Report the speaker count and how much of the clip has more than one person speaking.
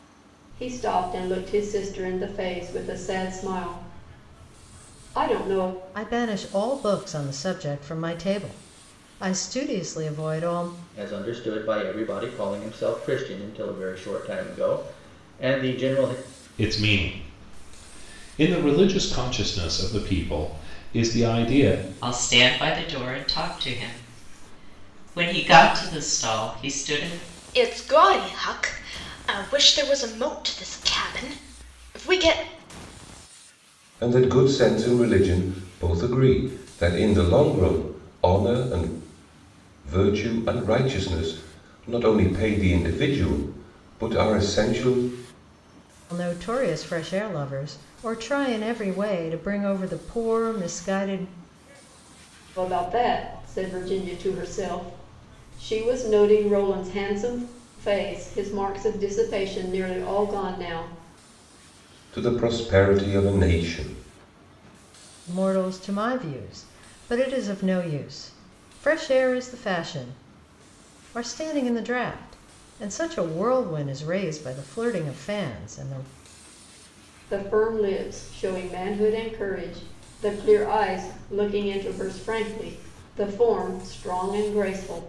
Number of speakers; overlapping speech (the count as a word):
seven, no overlap